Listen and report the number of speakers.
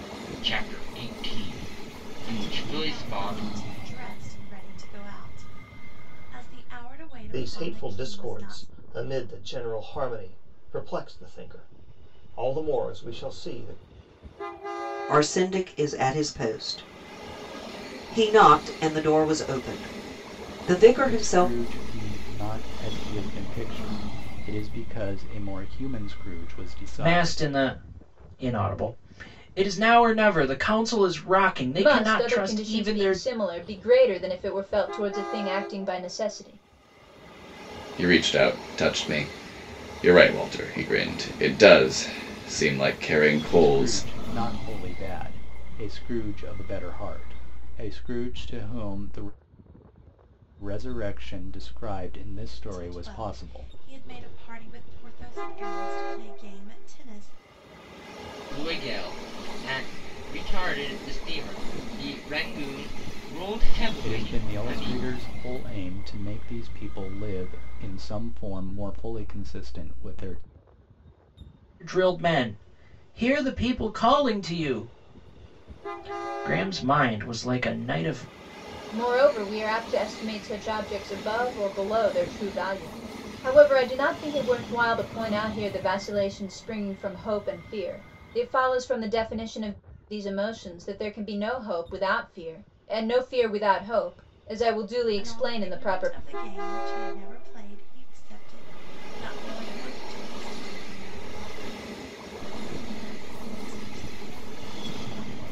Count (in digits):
8